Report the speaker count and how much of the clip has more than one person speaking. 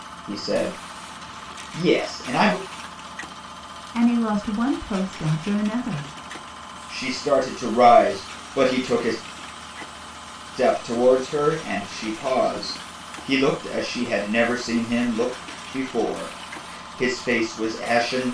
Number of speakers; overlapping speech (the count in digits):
2, no overlap